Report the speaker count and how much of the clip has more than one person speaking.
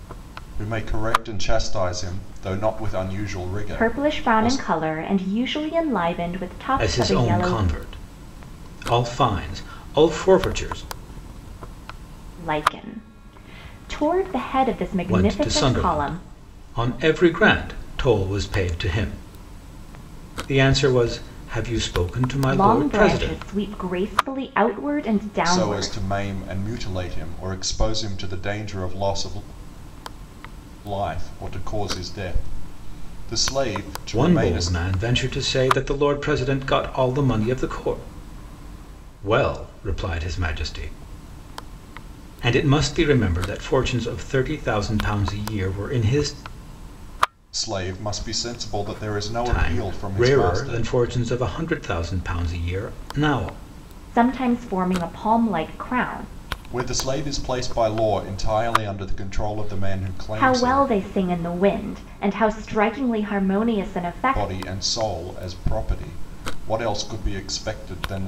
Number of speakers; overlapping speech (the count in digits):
3, about 11%